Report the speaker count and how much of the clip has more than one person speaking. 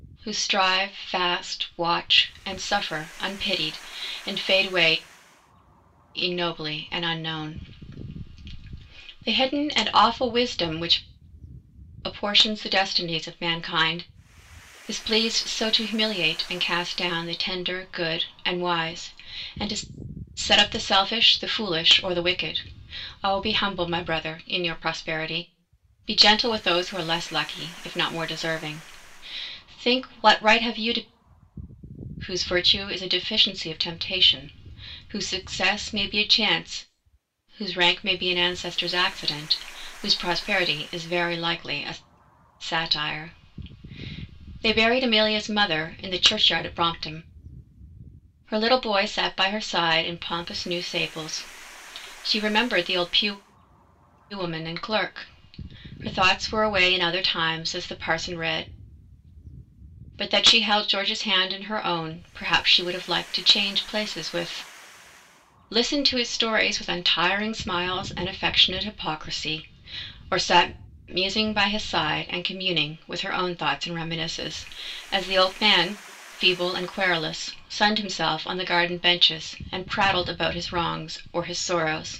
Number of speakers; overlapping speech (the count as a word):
one, no overlap